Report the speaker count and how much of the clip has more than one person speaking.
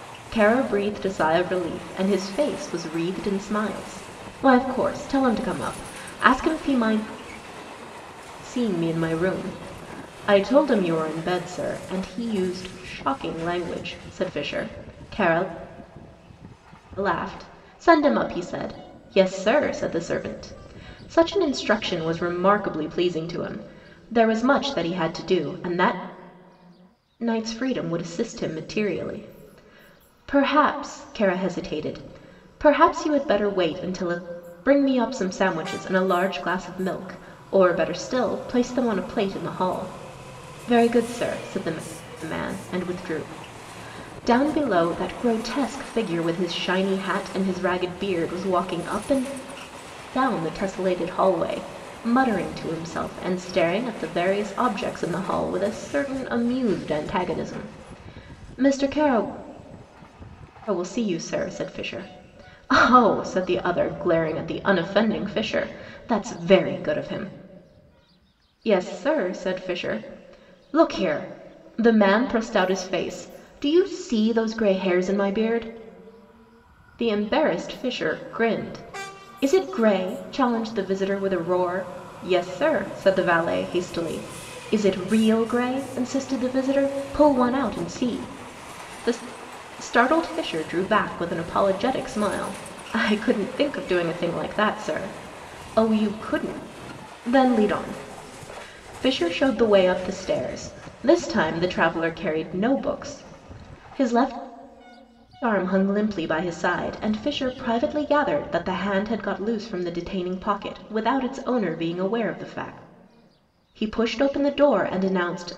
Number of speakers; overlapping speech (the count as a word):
one, no overlap